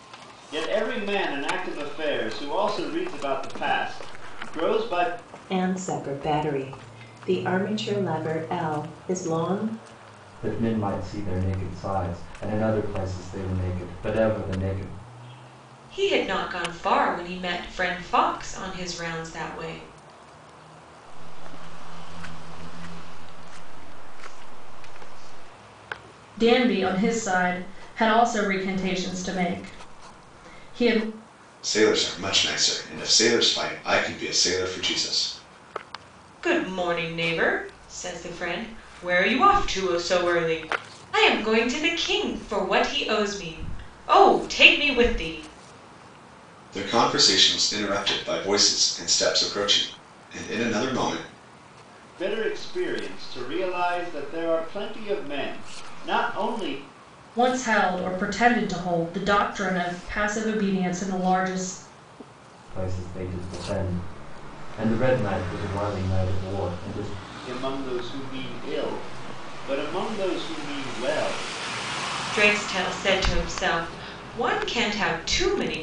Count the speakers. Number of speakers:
7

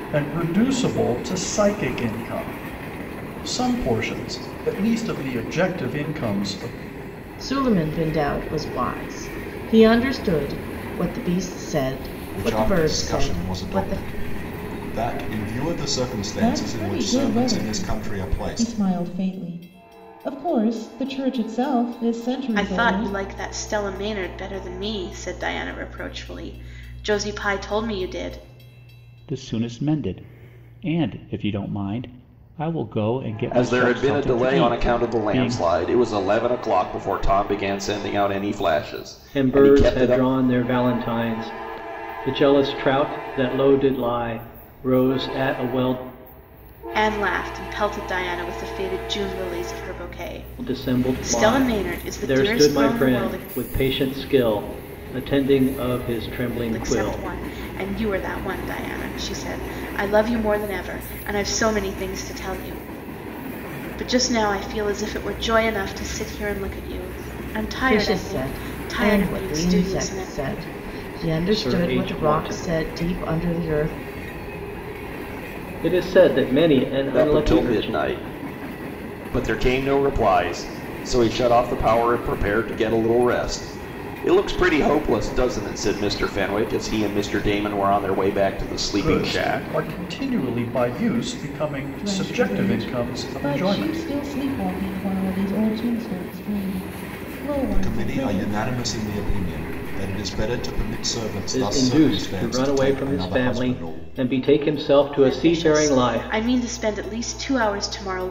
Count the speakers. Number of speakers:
8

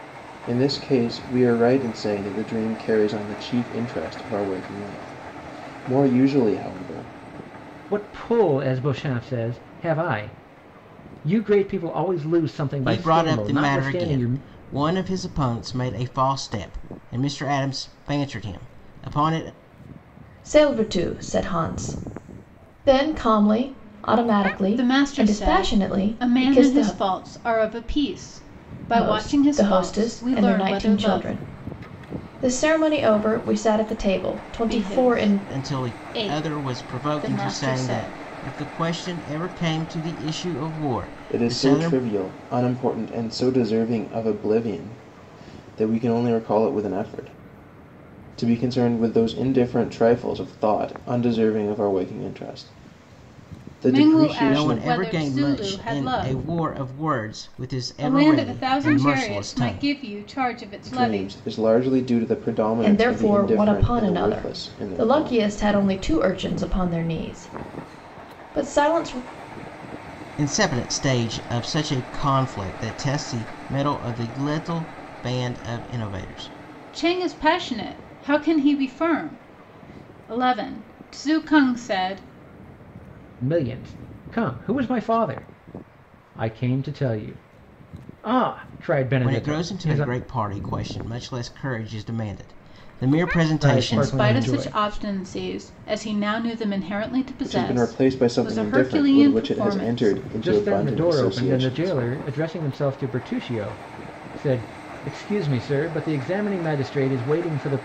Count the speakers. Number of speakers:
5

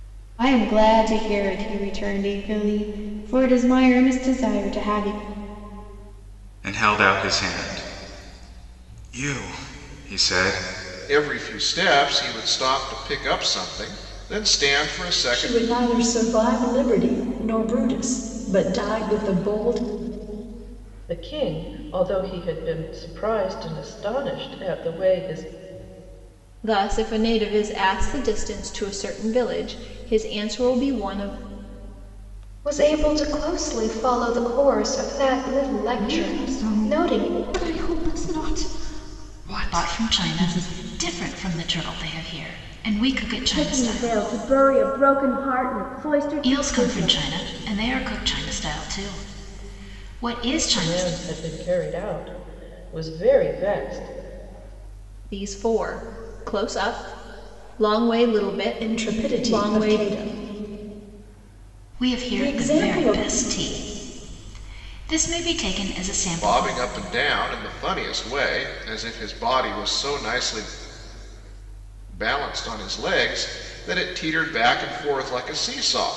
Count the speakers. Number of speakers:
10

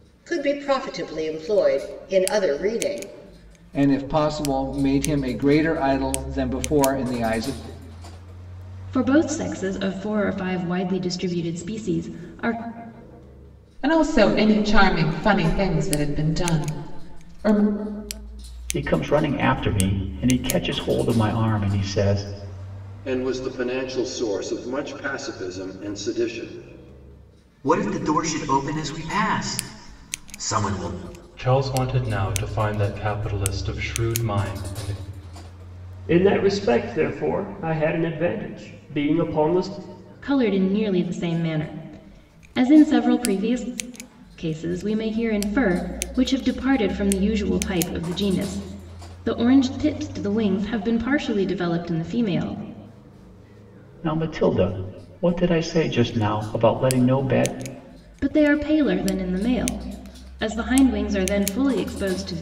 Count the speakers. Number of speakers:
9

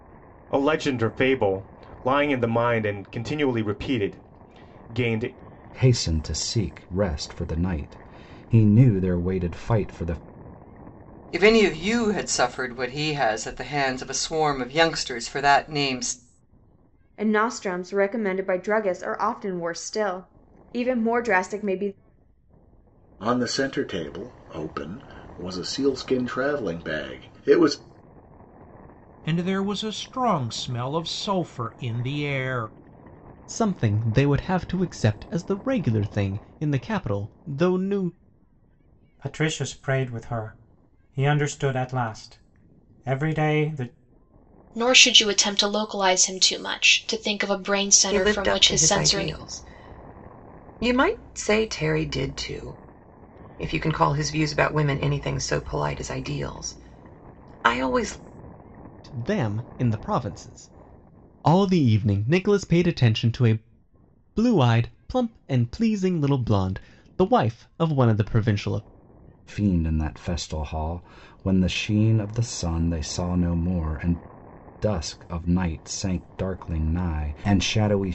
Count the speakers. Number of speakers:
10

